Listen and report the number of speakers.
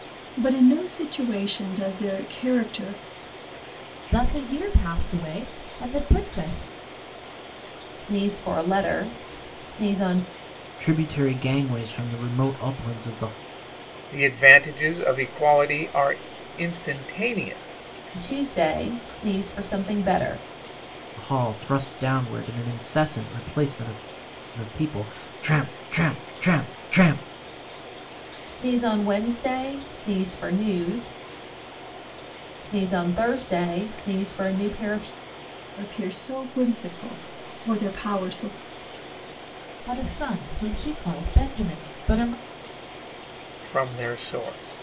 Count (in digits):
5